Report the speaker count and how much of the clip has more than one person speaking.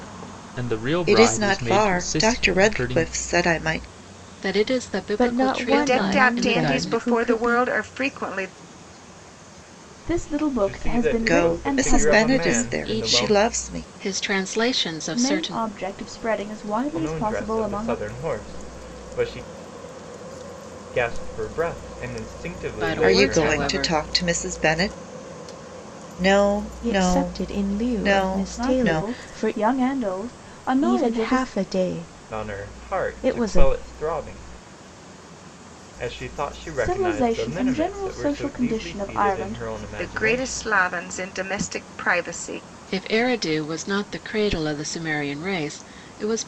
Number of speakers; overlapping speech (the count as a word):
seven, about 41%